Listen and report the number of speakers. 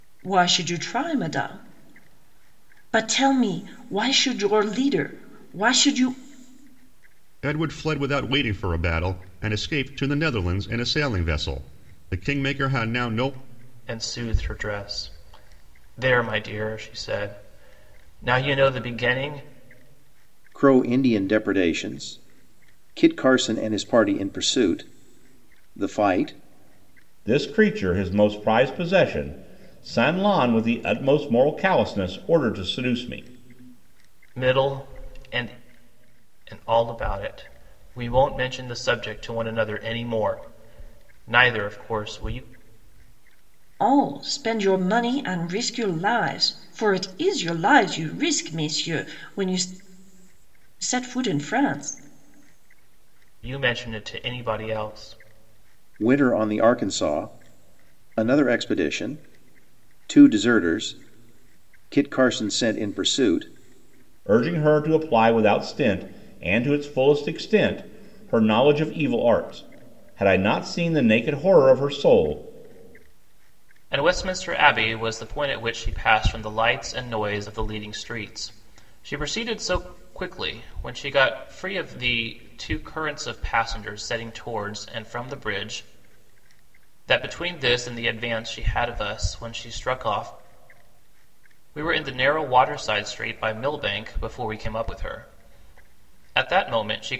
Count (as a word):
five